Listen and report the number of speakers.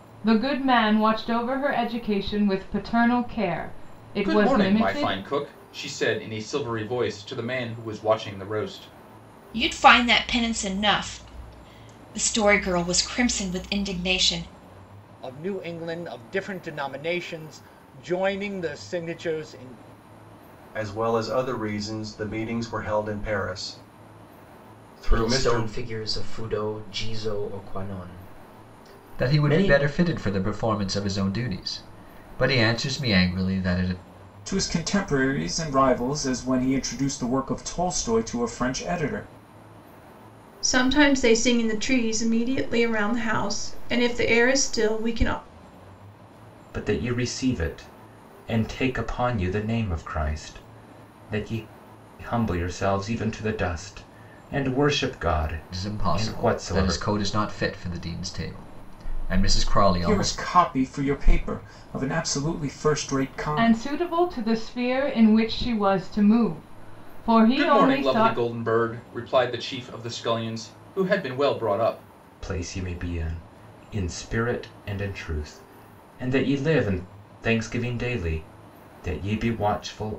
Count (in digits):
10